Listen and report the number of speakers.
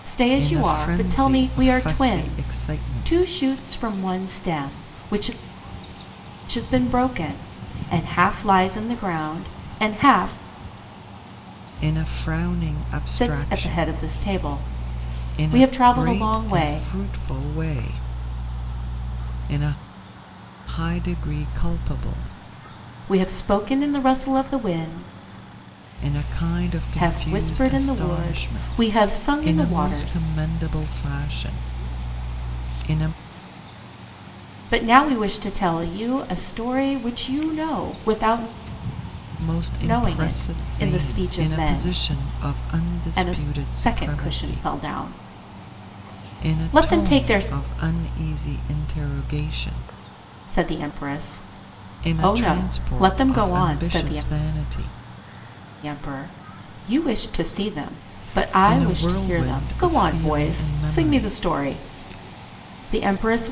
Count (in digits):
2